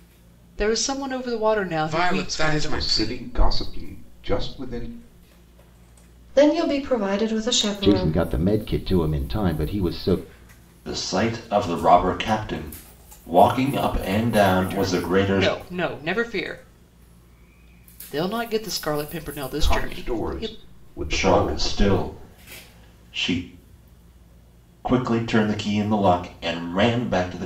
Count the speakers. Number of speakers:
six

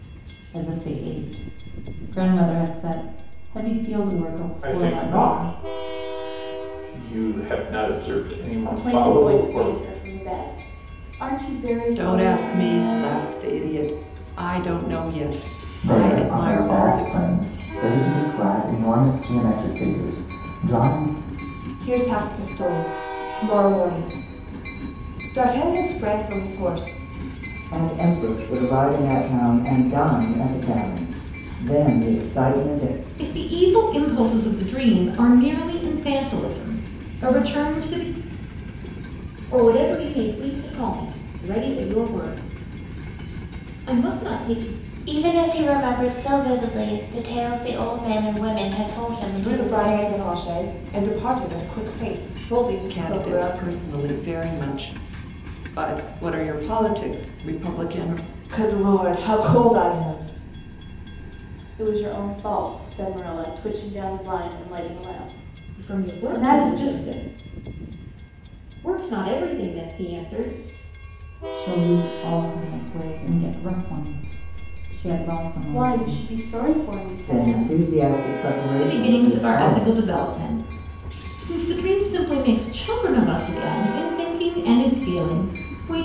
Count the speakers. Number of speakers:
ten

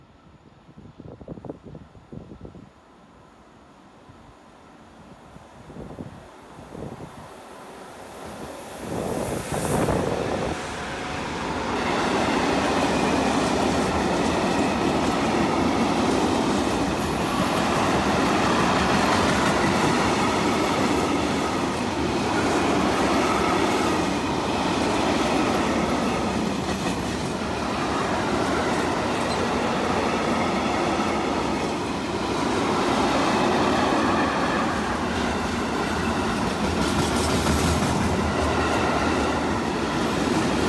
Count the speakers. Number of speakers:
zero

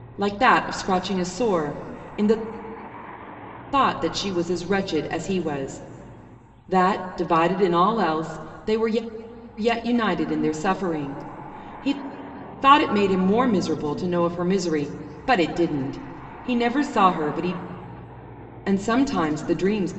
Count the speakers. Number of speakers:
one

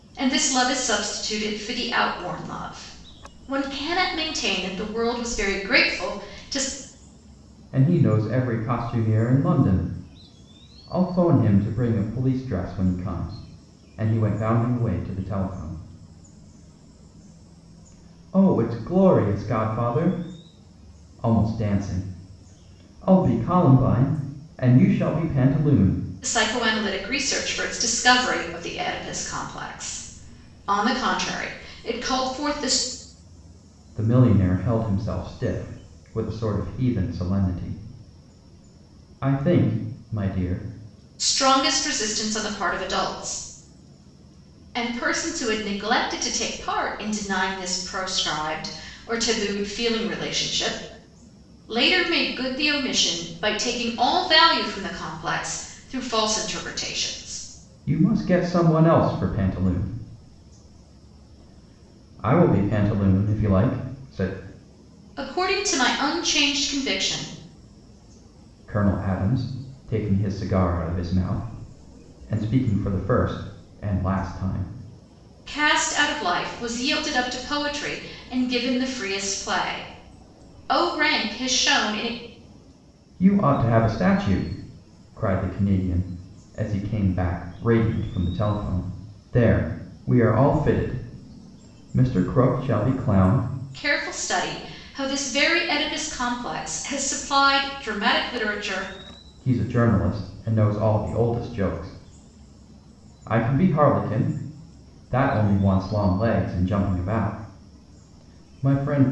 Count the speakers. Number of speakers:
two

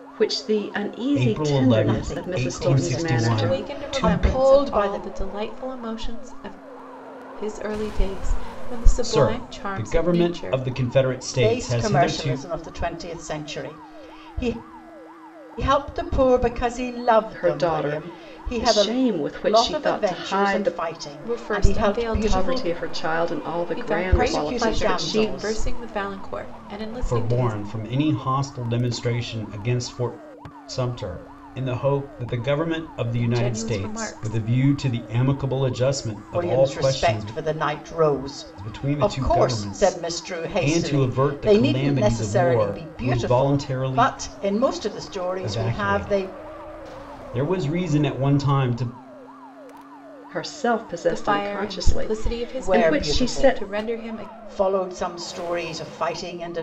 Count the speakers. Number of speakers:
four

